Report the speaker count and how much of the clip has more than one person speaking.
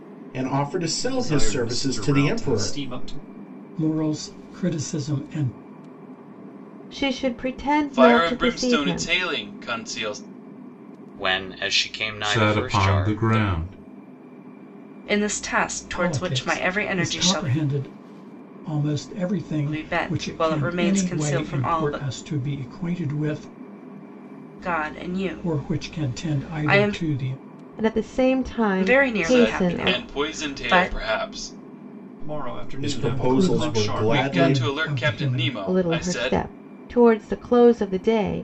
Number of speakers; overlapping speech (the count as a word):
eight, about 41%